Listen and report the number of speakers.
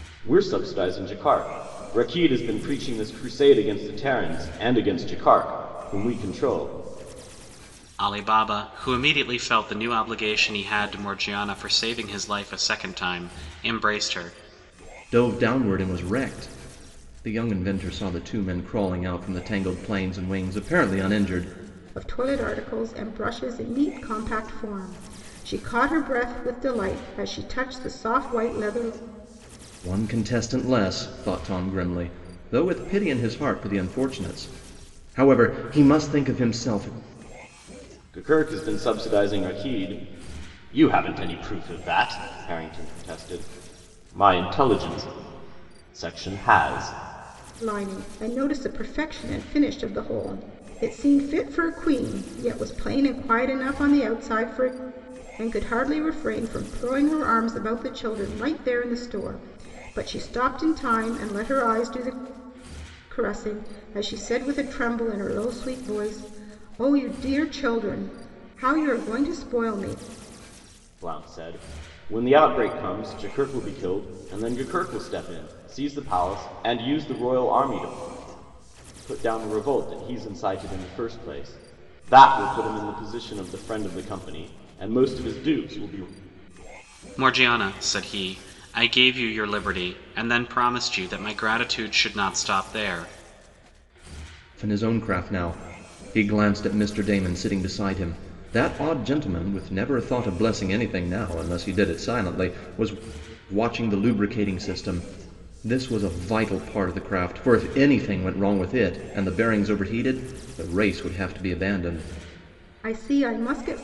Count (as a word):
four